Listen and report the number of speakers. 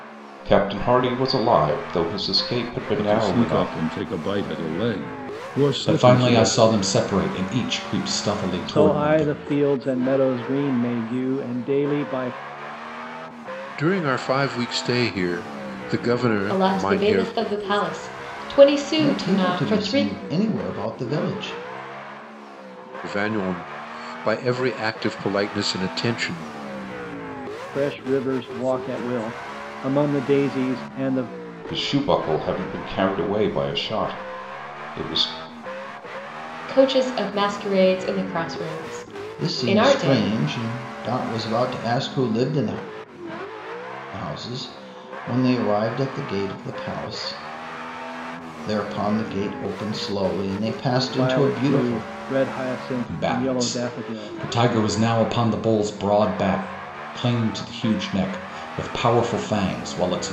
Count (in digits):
7